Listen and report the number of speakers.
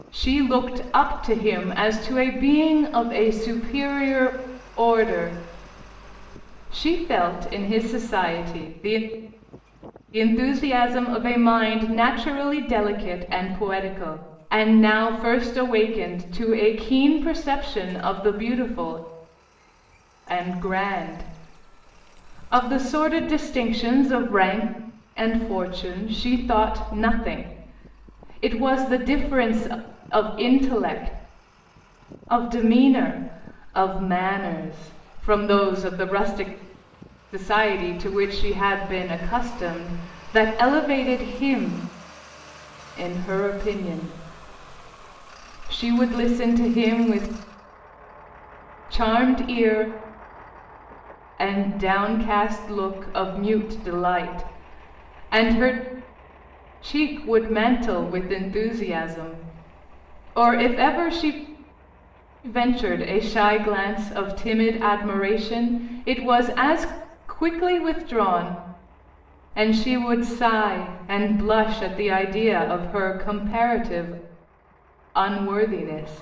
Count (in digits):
1